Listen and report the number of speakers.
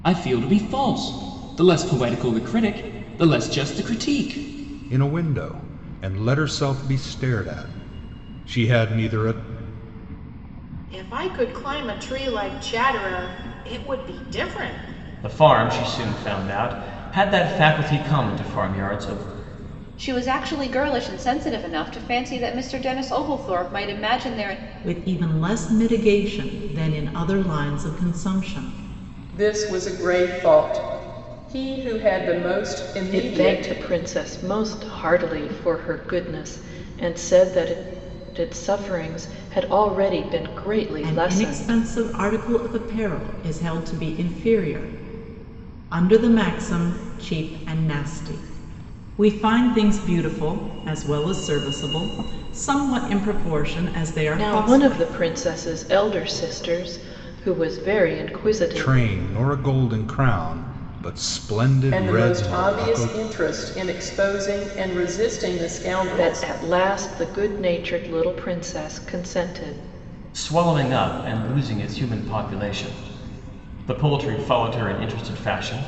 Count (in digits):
8